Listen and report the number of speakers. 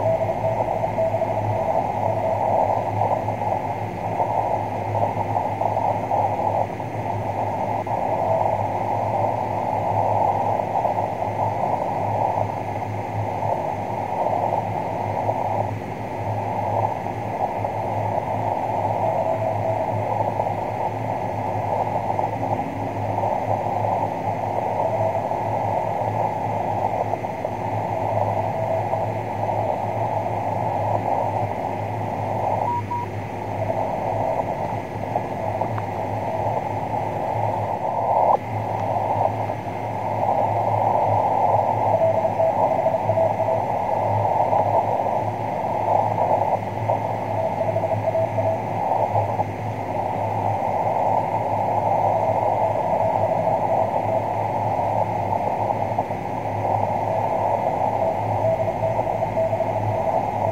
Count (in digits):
0